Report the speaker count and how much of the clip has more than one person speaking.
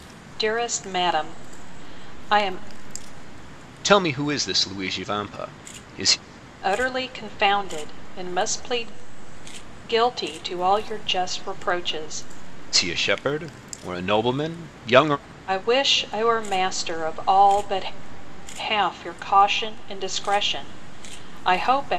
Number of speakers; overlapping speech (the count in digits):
2, no overlap